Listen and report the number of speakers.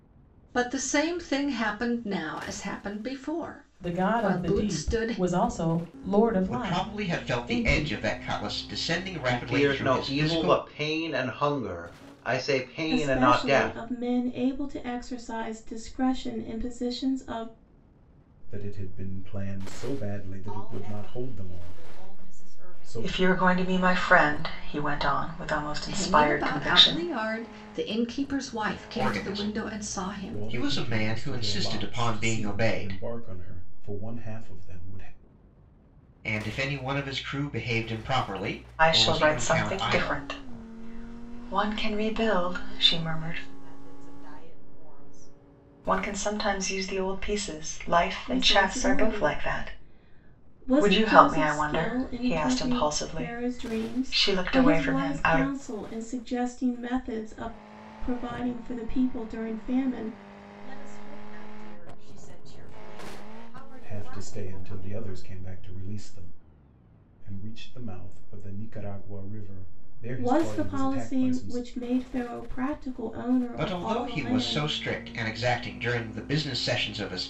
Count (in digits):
8